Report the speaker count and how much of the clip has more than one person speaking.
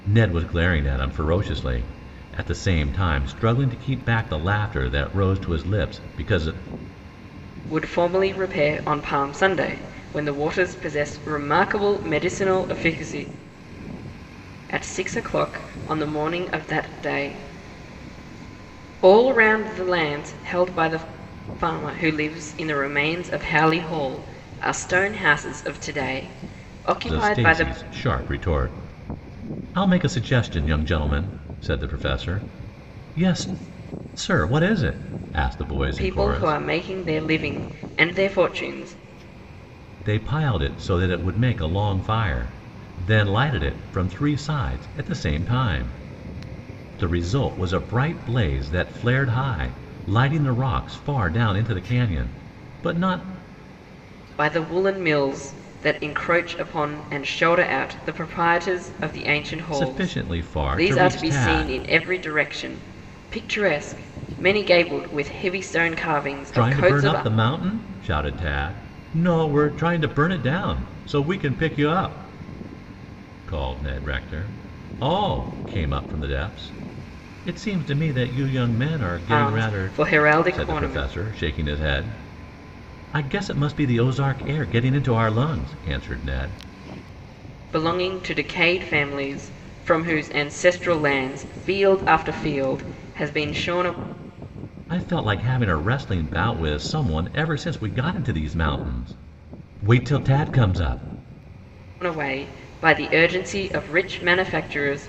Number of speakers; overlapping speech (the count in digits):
2, about 5%